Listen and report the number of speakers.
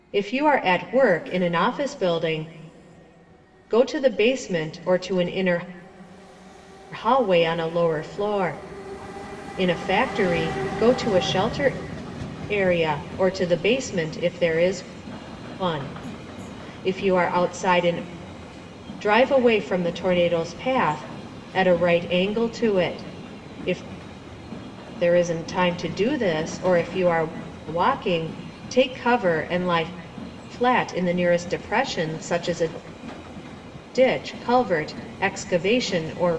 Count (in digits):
1